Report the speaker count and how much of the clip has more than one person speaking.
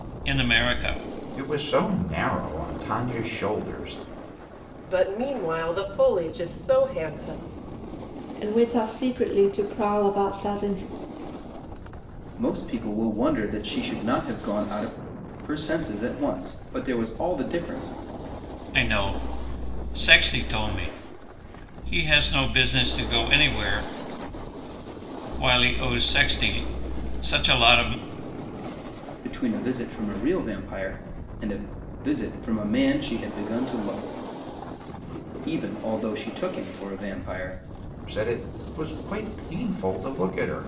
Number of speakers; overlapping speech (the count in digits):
5, no overlap